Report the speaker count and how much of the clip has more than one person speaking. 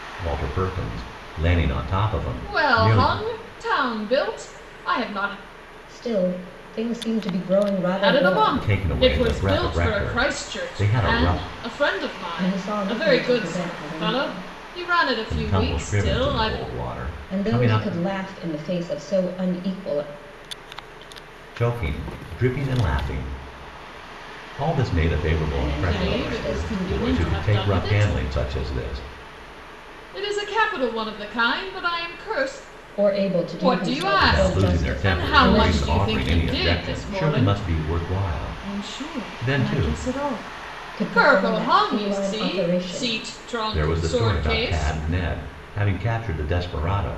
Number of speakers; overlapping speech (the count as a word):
three, about 44%